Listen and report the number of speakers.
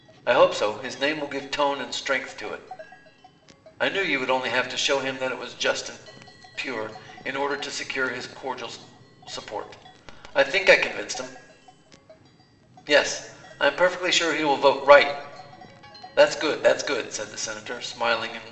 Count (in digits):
1